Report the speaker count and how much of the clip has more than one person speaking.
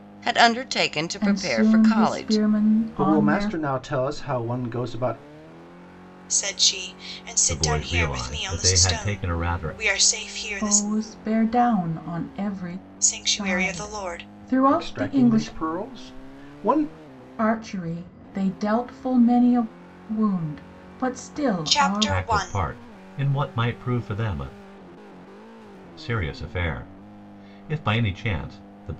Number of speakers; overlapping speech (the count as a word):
five, about 26%